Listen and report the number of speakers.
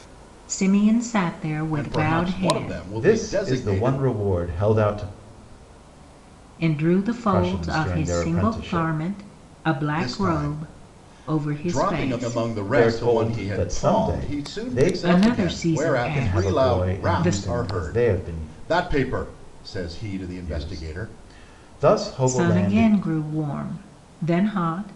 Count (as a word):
three